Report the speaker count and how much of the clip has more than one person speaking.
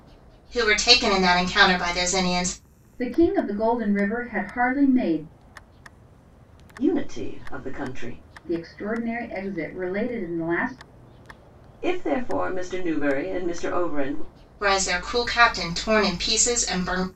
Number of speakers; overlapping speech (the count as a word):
three, no overlap